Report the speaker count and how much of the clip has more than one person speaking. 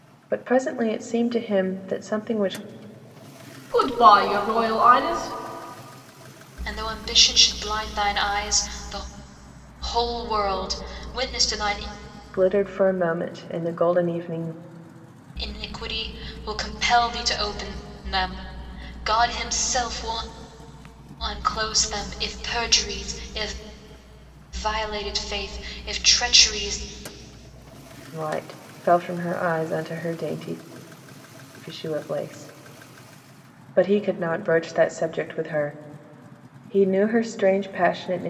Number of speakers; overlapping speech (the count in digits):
3, no overlap